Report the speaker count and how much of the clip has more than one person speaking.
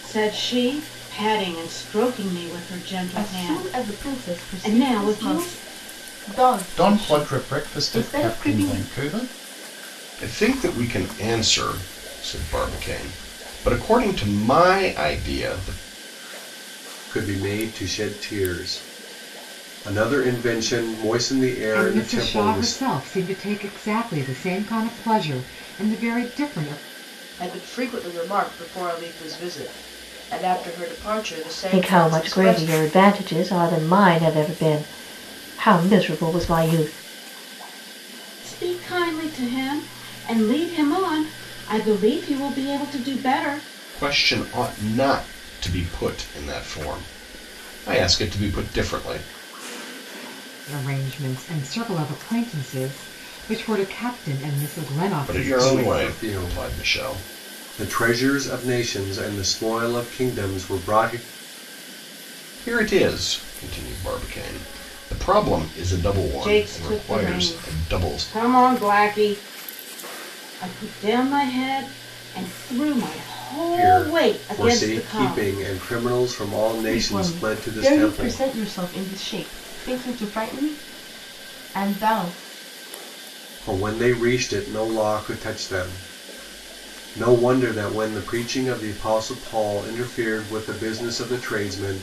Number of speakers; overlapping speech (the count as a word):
eight, about 15%